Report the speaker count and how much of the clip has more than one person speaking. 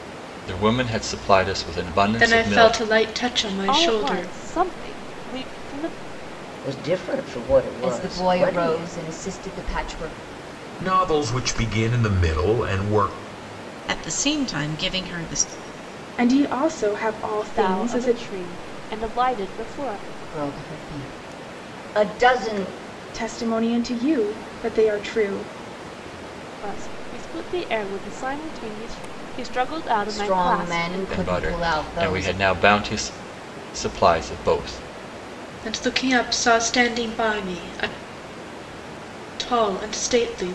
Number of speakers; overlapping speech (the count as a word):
eight, about 15%